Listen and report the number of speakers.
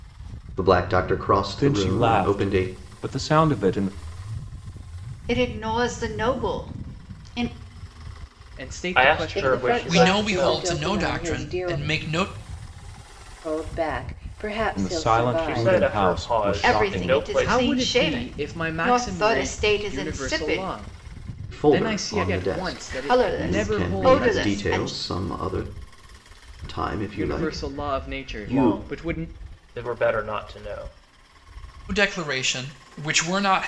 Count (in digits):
7